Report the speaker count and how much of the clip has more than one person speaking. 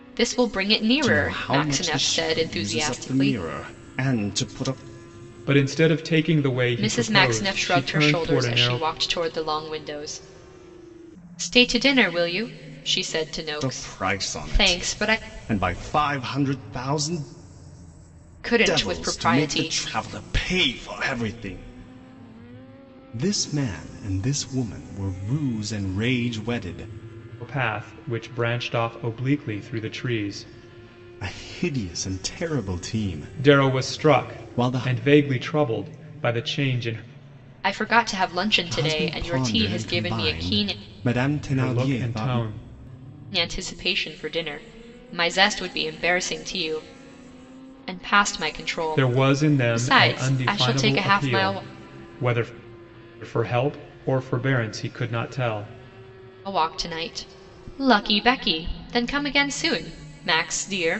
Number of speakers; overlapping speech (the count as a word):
three, about 24%